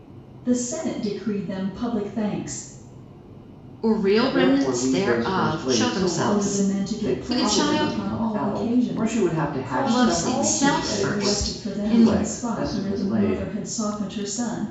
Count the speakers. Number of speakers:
3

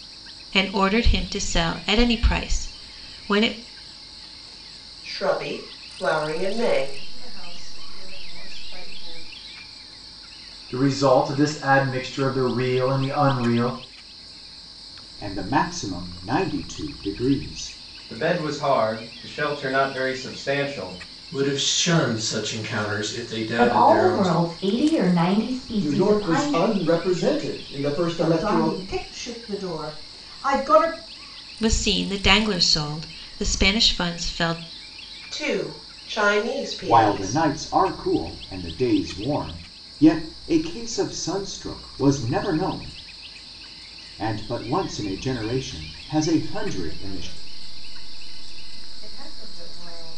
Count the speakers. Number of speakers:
10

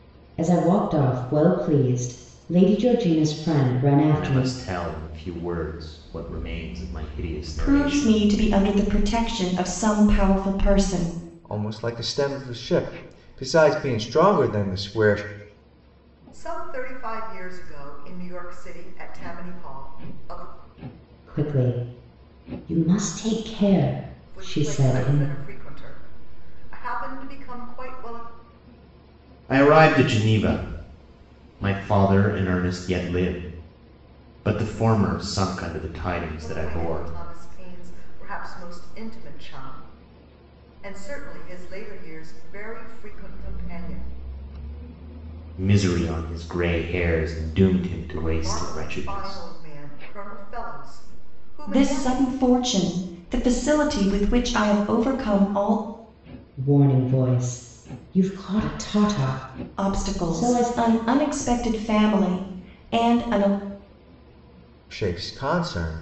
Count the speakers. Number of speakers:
5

